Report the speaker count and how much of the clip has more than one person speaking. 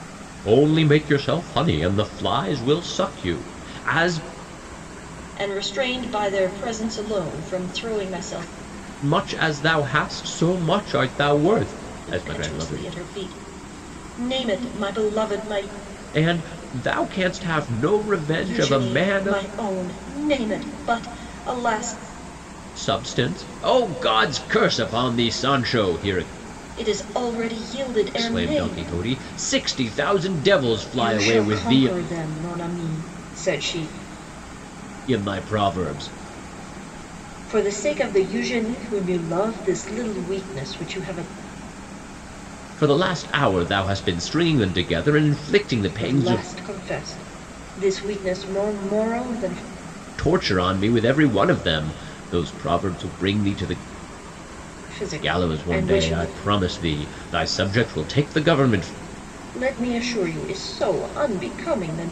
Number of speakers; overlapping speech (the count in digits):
2, about 9%